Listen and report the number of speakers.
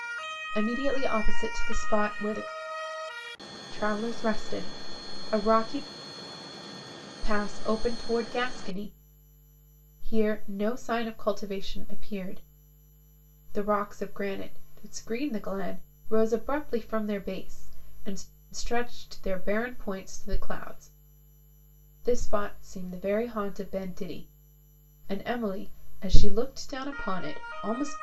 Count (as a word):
one